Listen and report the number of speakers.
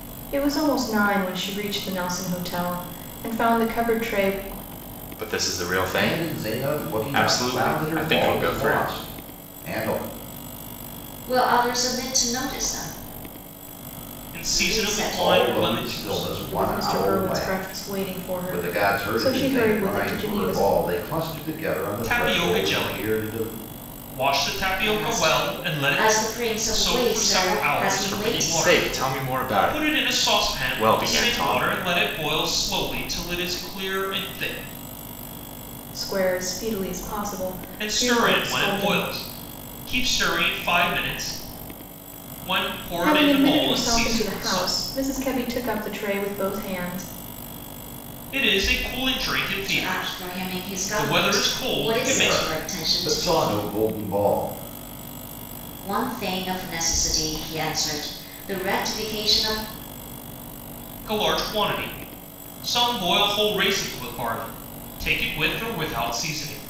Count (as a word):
five